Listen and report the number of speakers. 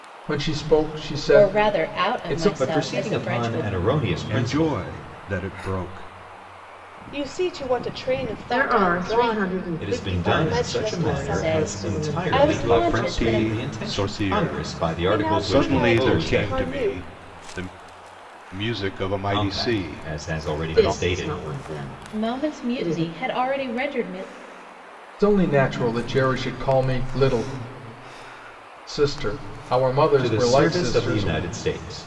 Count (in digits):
6